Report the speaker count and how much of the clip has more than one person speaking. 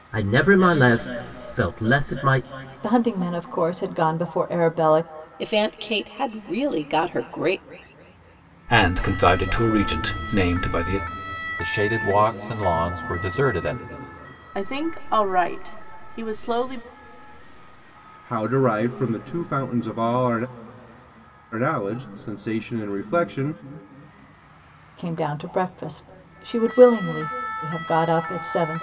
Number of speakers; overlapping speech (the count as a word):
seven, no overlap